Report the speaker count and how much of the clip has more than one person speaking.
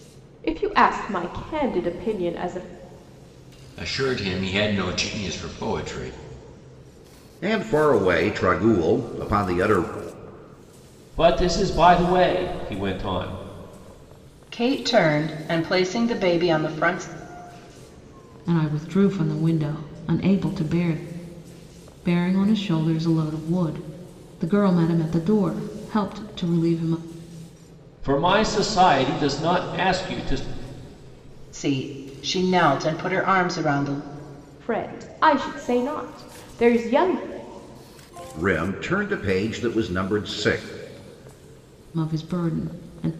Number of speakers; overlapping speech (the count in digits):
6, no overlap